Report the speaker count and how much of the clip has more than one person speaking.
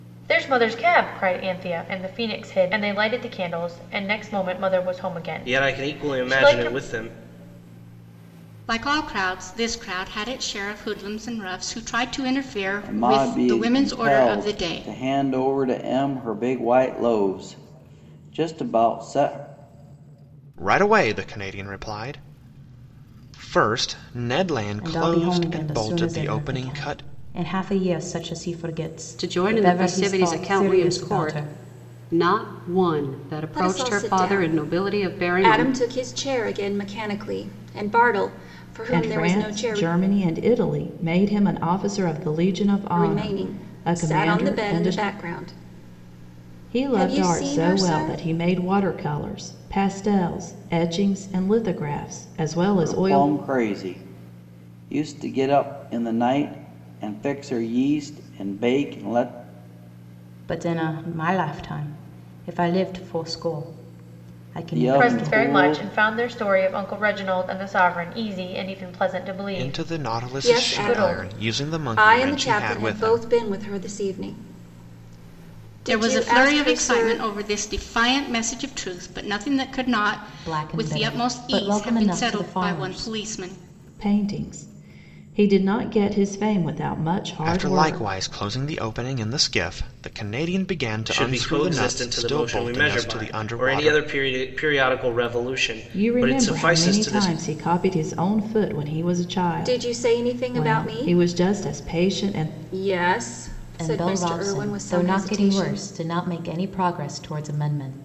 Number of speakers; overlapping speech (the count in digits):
9, about 32%